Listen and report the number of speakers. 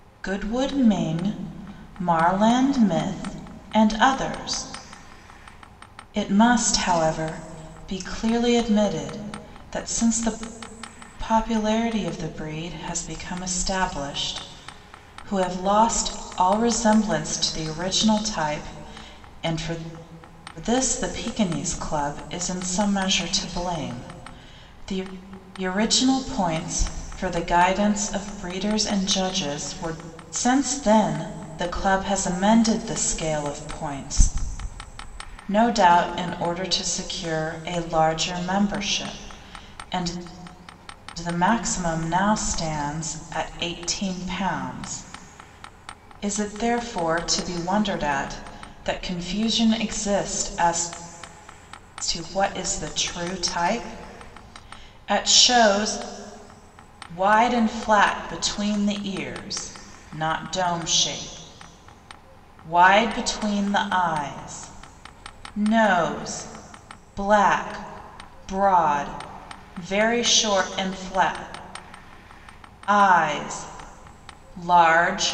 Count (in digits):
1